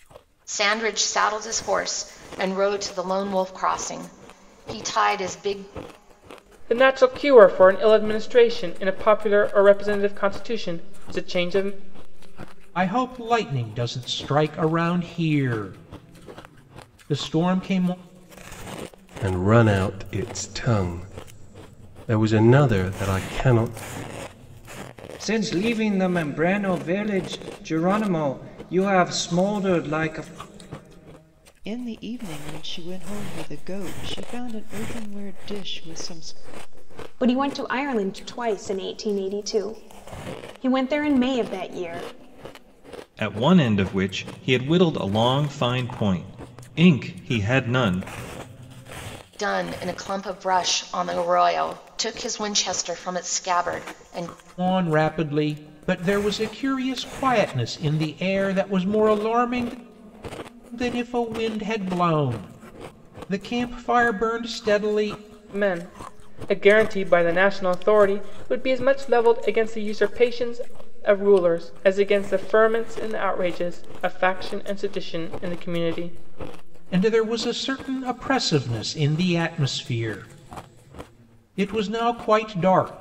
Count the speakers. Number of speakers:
eight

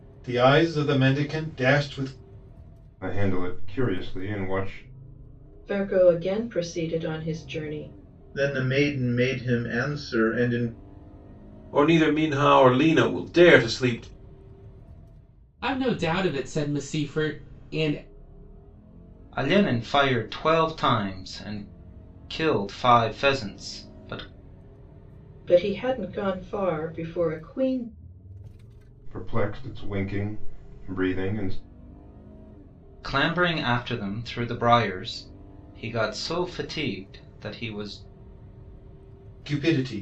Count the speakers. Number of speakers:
seven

